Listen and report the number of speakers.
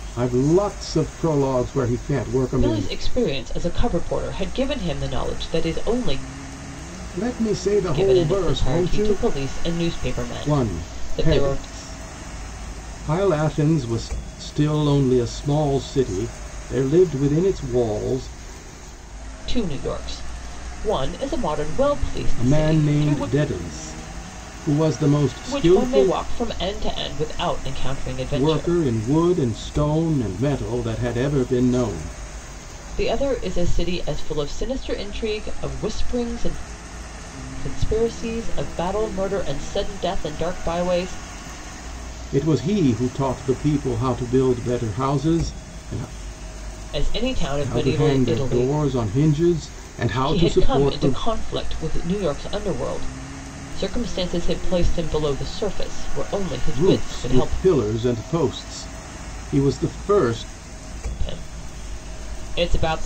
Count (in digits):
2